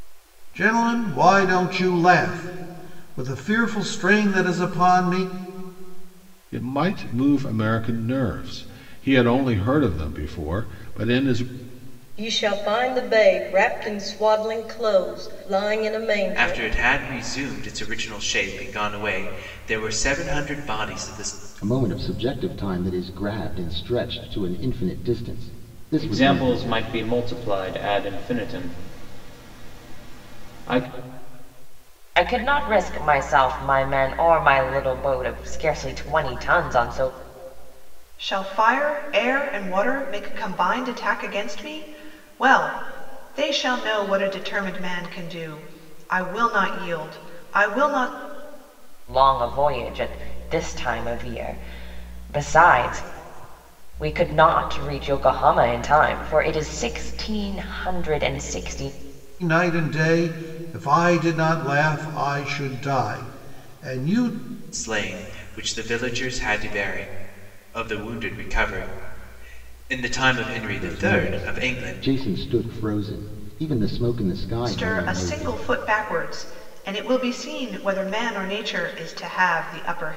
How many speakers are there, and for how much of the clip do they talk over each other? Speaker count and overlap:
8, about 4%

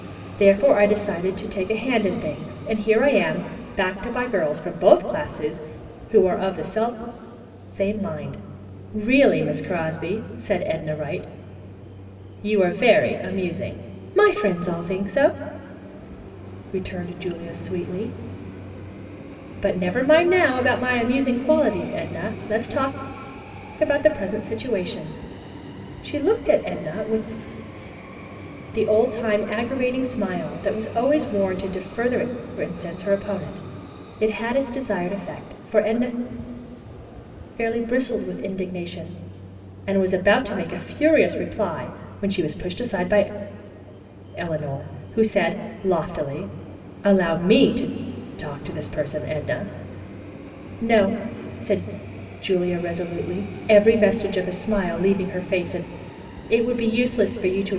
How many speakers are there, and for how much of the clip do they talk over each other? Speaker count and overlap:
1, no overlap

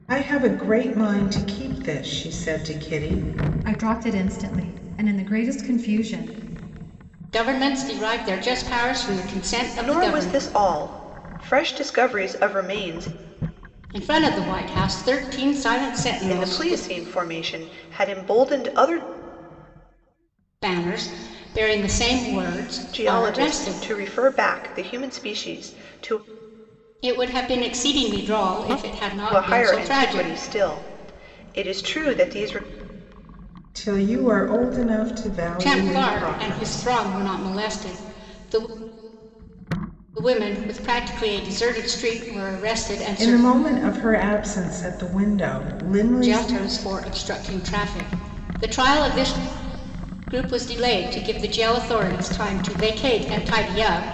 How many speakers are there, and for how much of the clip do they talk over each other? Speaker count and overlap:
4, about 10%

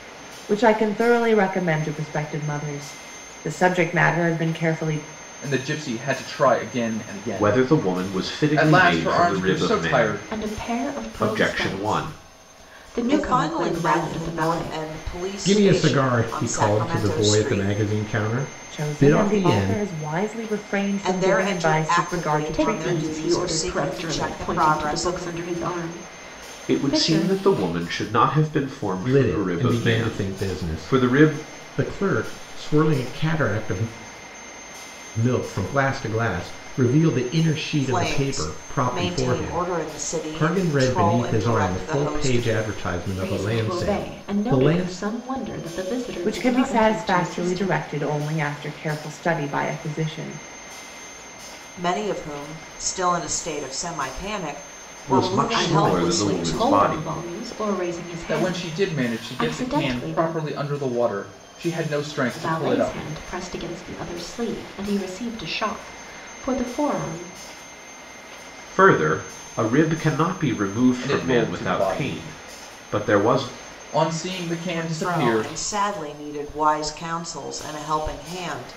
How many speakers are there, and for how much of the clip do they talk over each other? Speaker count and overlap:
6, about 42%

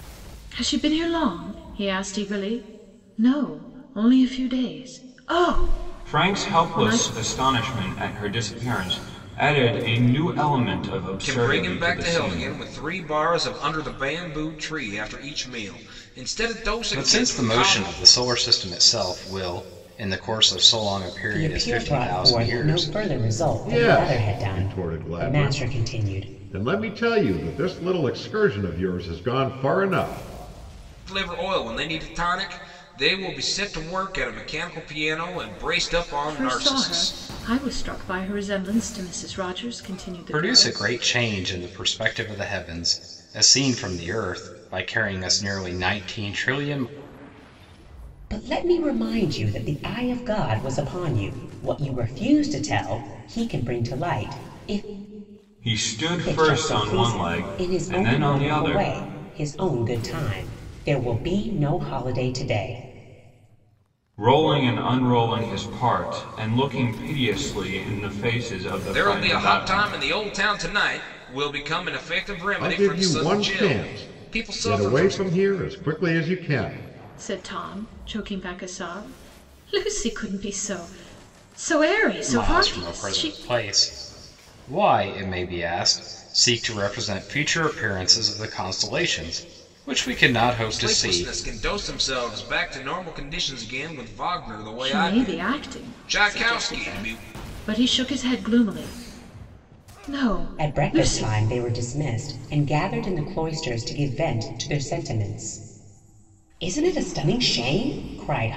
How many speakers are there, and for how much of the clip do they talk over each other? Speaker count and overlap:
6, about 19%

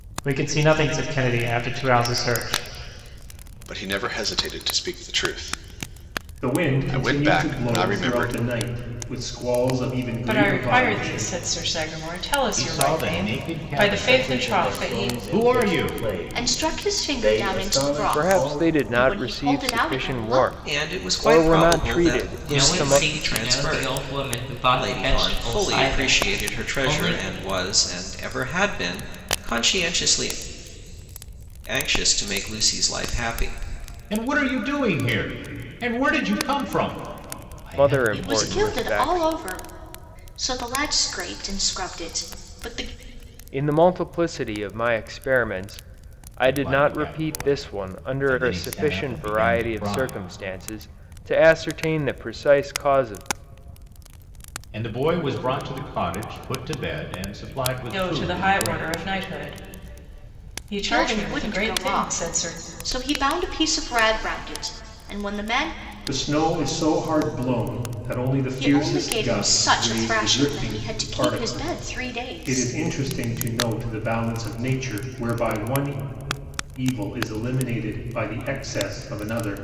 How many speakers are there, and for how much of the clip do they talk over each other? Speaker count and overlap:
10, about 38%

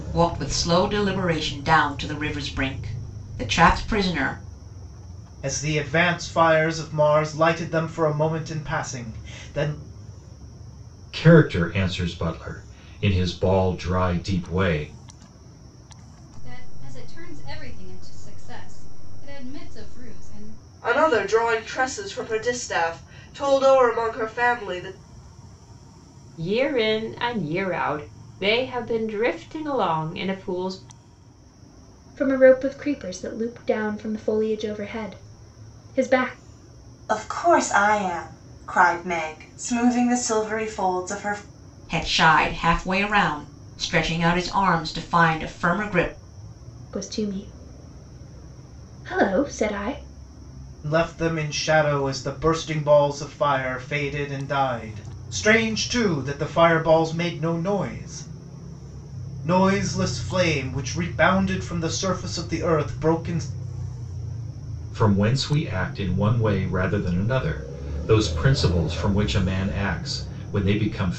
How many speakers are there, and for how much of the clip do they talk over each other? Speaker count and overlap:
8, no overlap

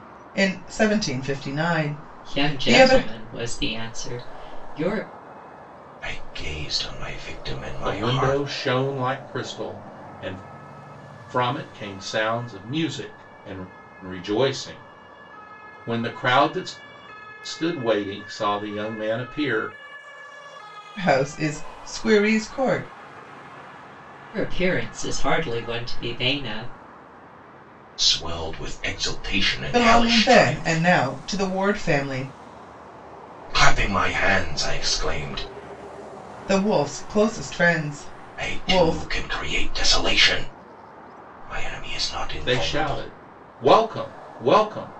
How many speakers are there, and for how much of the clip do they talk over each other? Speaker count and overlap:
4, about 9%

